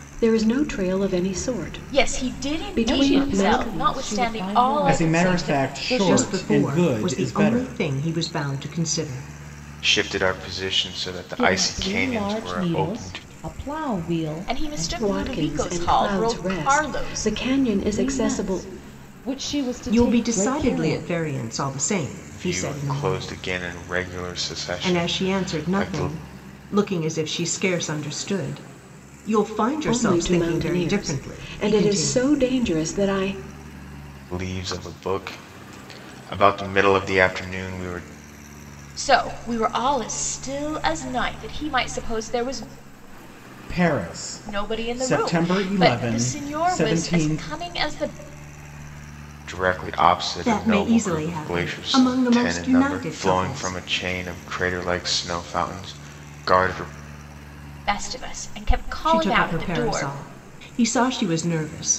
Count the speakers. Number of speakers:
six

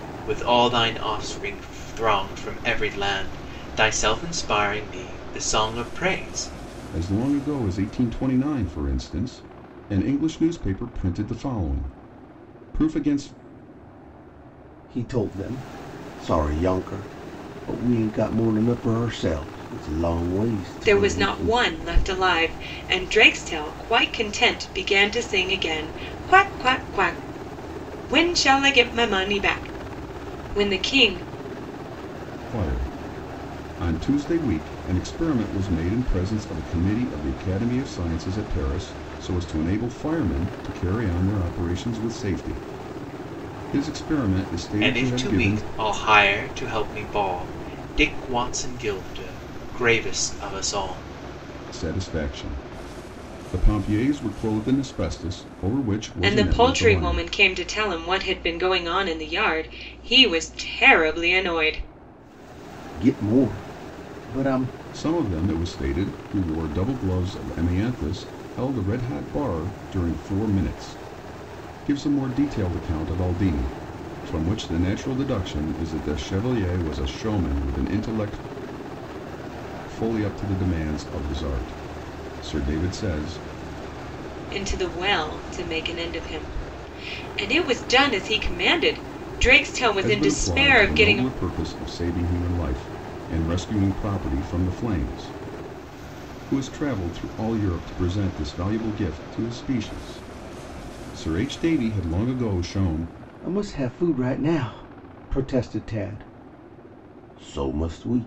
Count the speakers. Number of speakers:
four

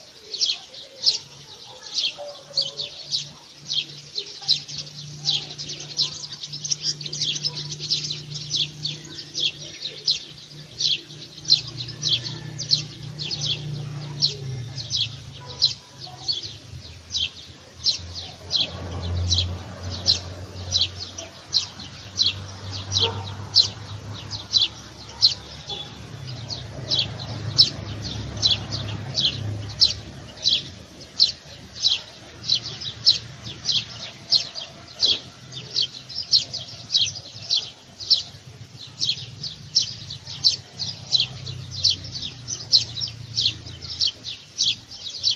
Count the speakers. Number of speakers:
zero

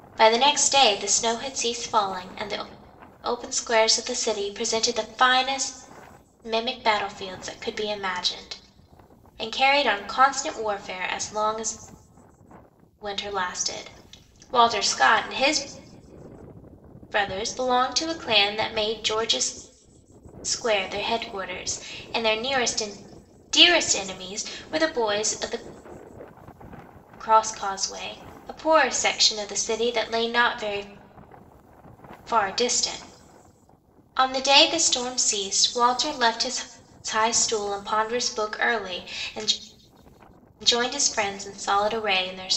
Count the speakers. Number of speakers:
one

